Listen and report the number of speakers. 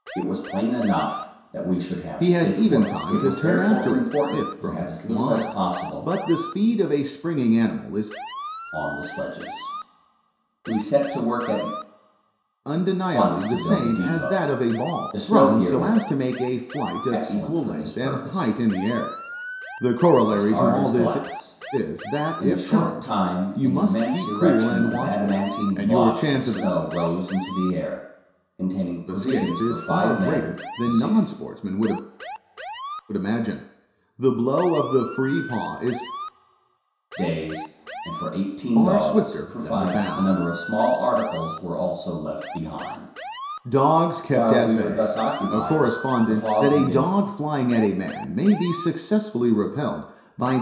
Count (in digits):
2